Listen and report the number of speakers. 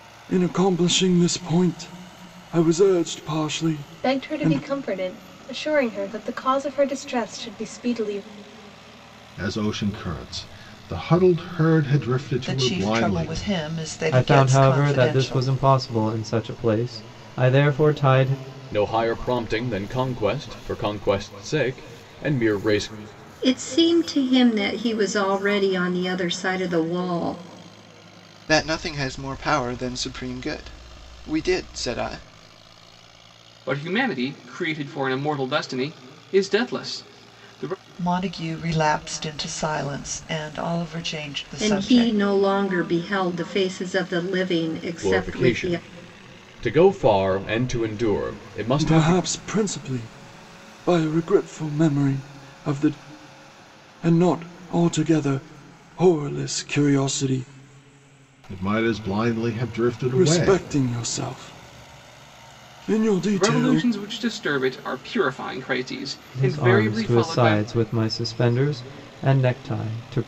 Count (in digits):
9